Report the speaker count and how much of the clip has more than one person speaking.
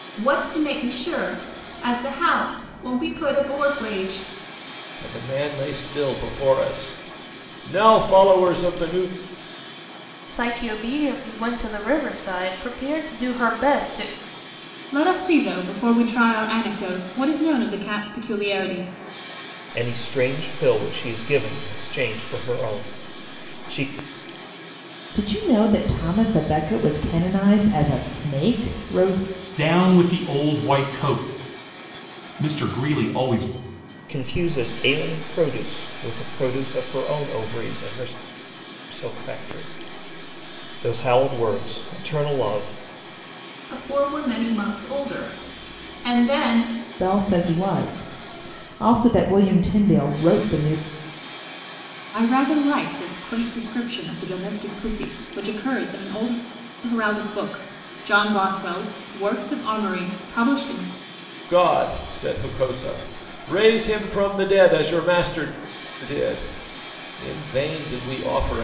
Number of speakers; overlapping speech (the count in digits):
7, no overlap